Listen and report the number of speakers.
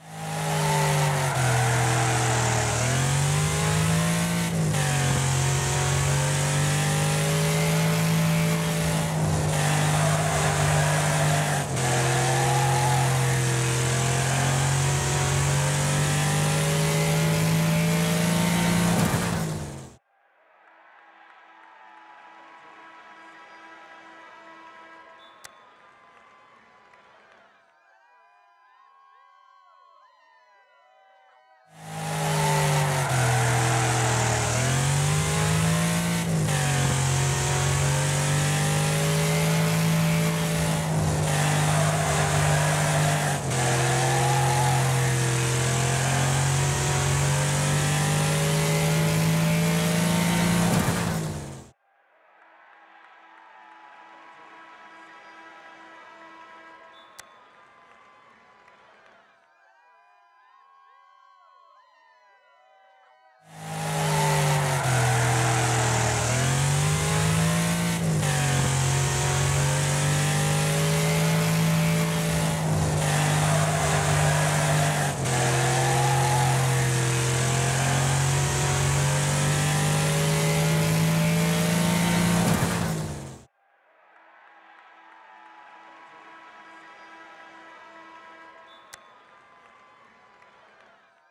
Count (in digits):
0